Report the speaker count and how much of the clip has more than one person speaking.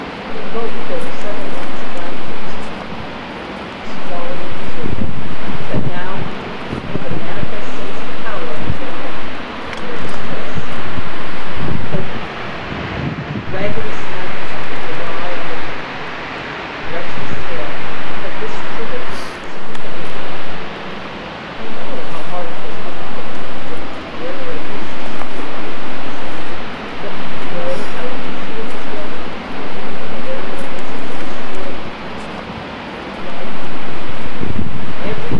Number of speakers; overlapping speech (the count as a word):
one, no overlap